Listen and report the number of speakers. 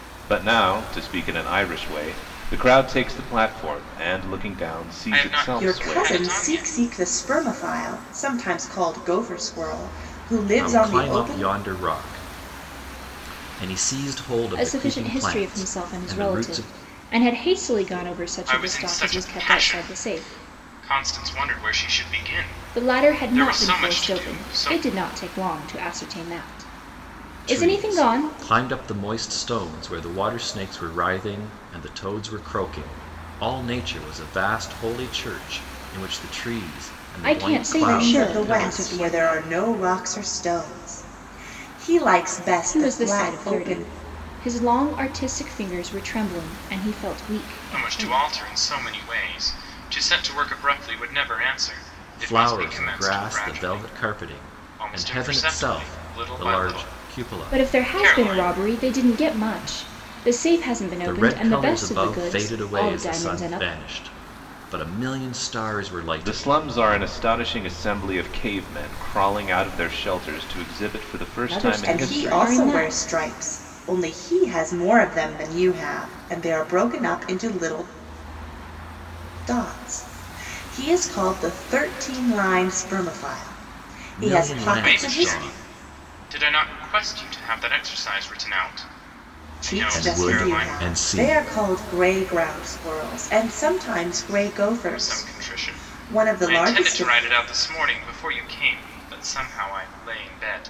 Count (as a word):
five